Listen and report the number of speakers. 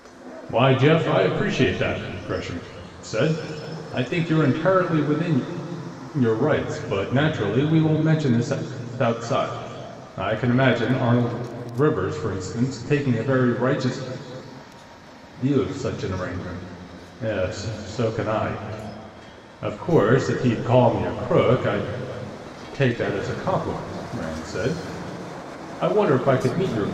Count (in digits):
1